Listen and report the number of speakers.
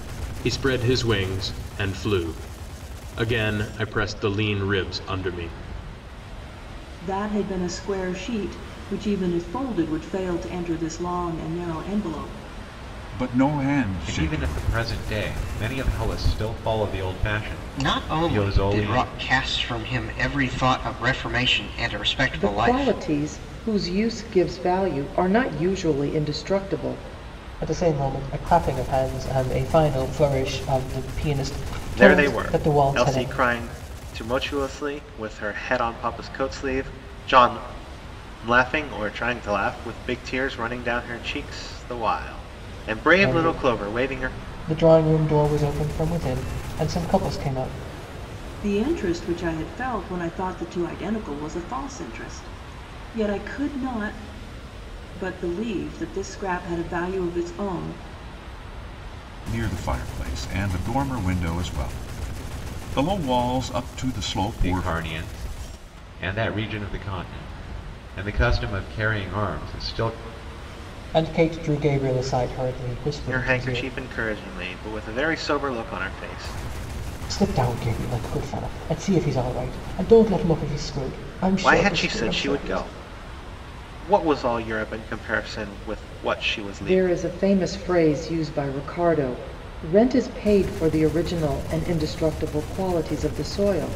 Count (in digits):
8